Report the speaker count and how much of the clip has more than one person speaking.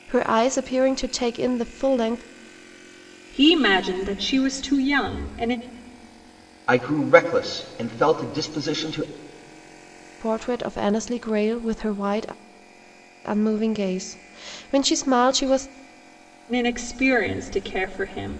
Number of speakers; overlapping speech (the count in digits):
3, no overlap